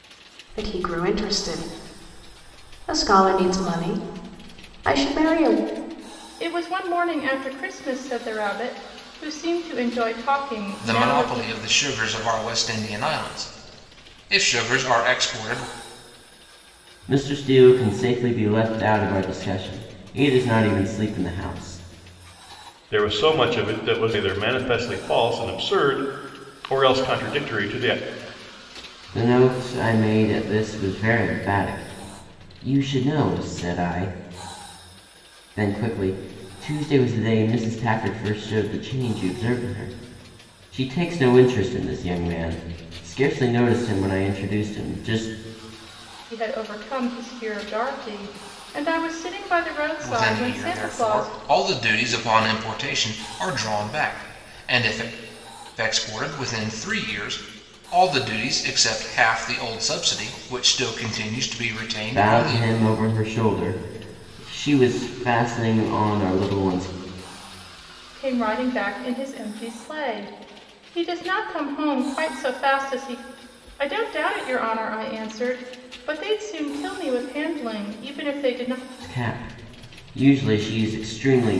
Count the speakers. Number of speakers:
5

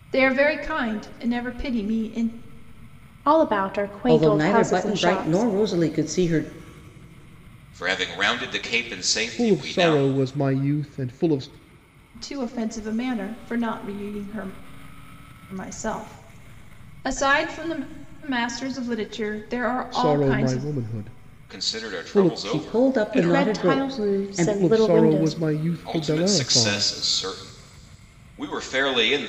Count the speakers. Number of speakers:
5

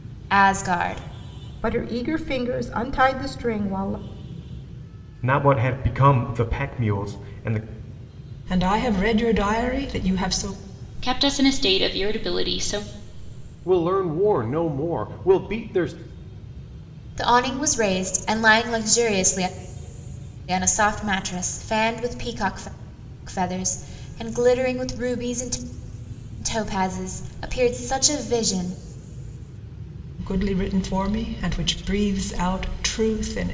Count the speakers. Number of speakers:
6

